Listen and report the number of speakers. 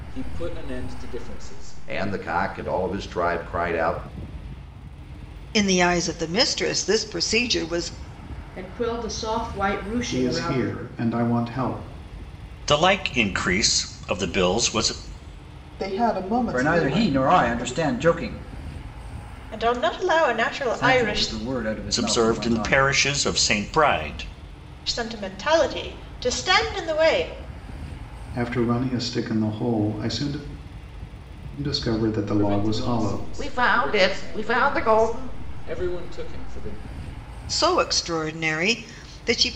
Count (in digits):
9